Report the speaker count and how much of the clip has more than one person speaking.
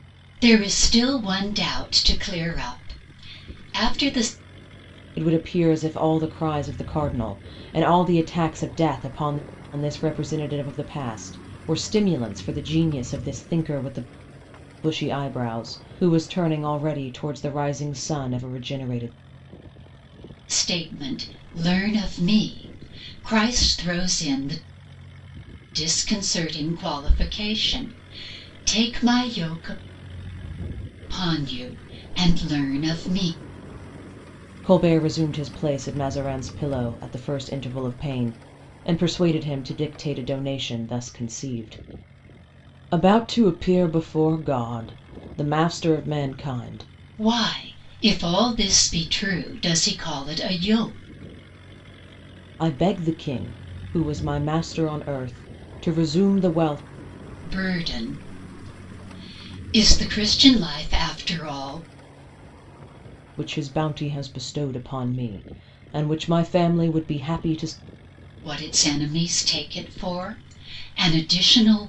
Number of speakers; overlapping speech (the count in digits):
2, no overlap